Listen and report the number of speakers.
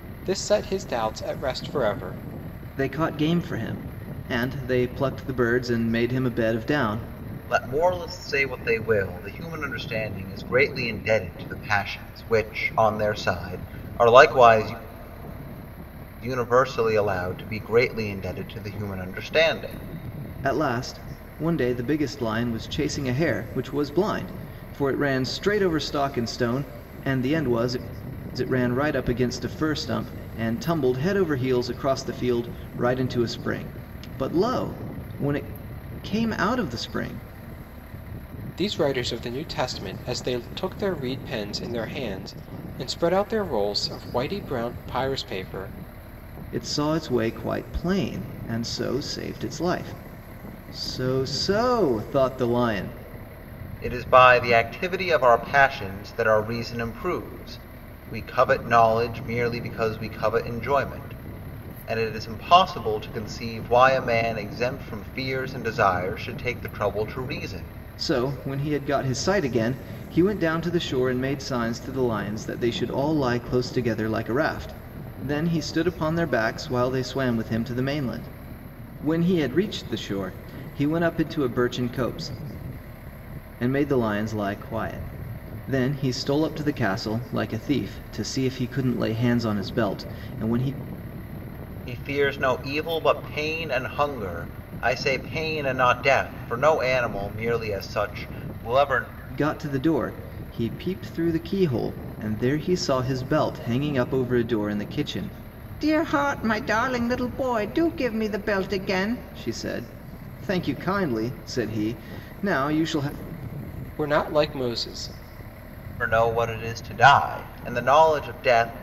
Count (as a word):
three